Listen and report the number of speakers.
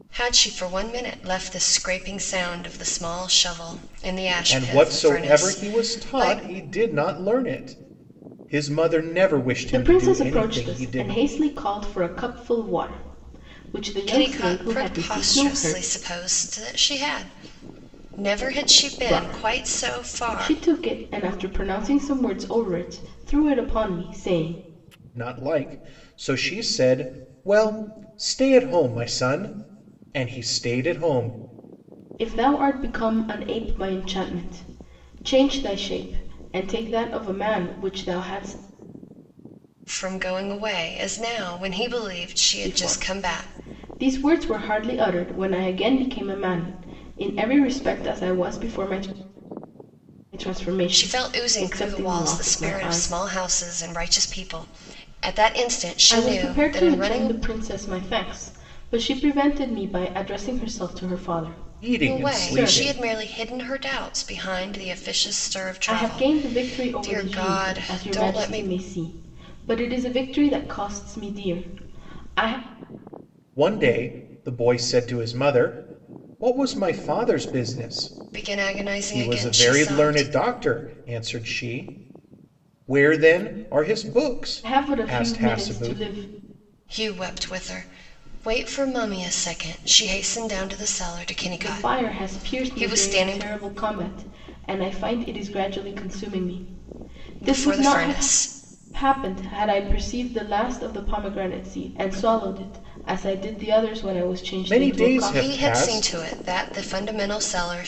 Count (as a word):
three